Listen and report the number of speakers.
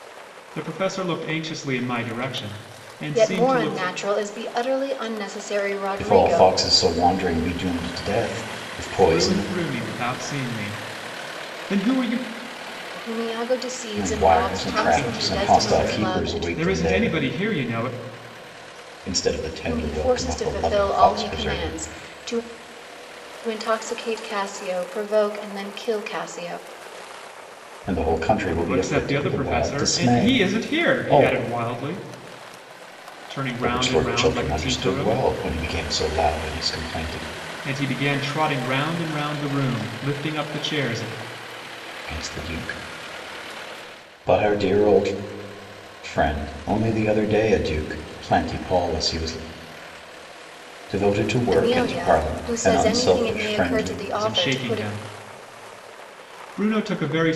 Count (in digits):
3